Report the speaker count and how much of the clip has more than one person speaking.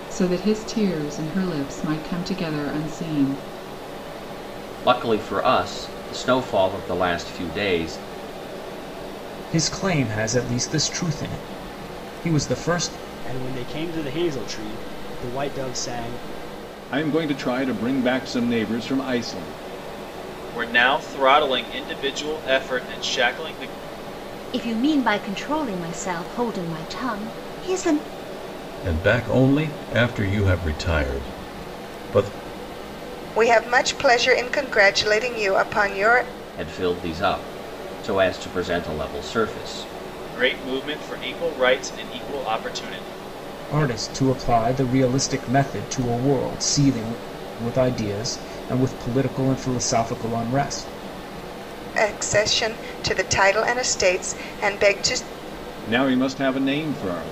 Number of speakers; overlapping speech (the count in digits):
9, no overlap